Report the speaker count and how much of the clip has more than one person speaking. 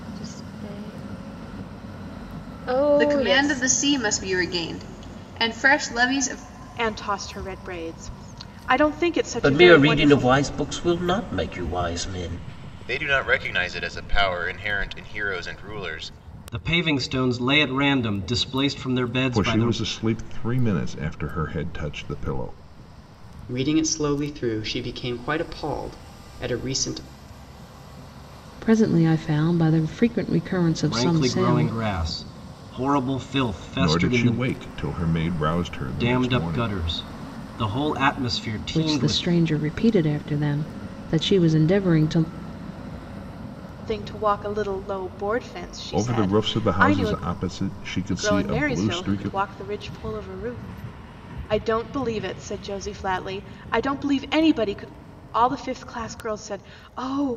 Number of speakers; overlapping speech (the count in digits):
9, about 14%